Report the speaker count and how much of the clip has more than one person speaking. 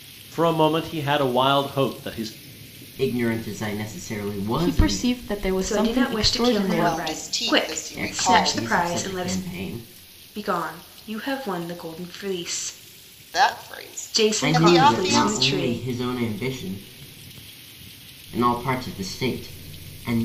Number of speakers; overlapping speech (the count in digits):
5, about 30%